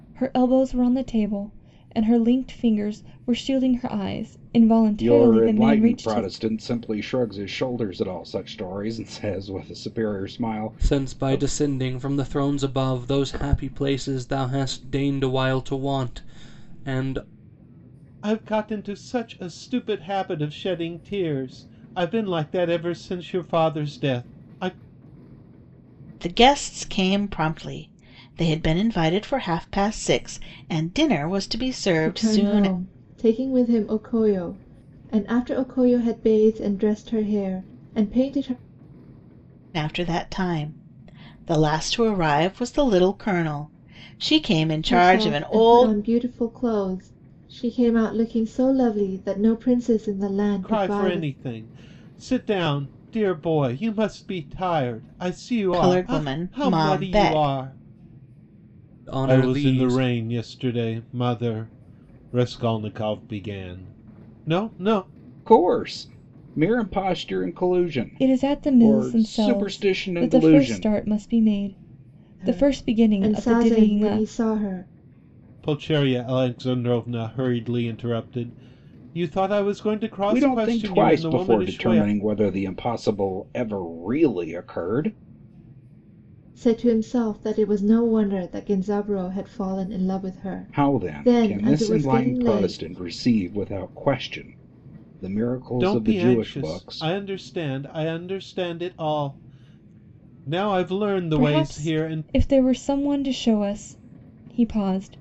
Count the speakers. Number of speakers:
6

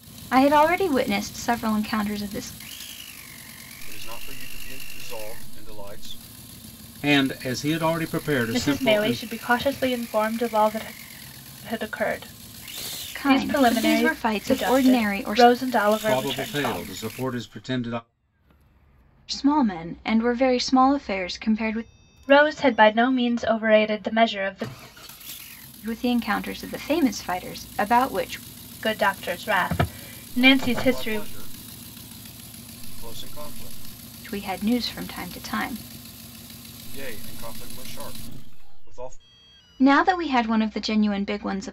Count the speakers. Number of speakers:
4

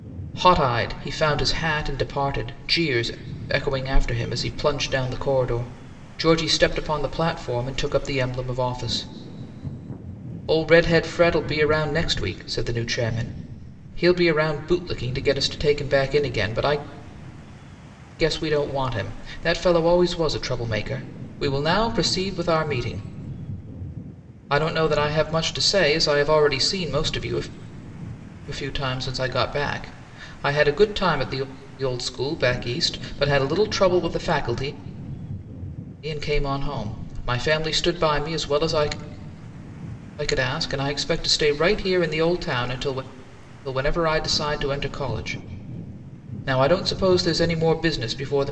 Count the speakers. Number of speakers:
1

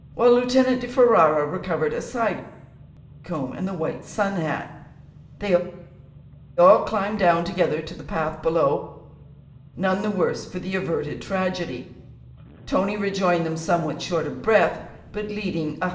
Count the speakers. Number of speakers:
1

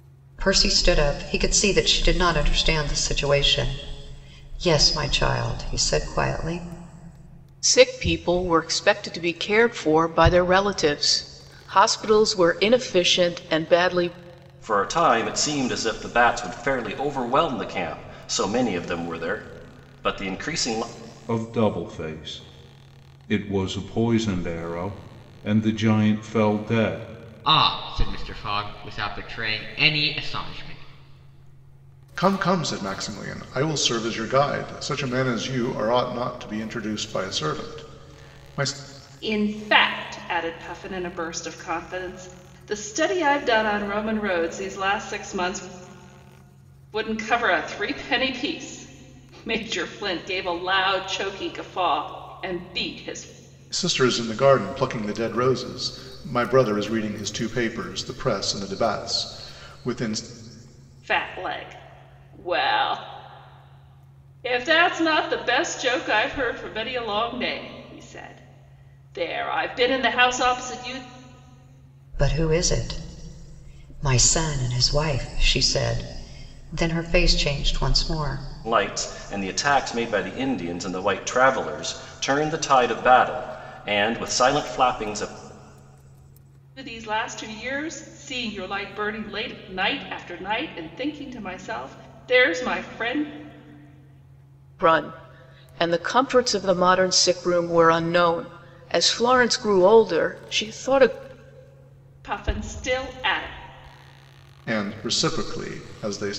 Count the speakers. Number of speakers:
7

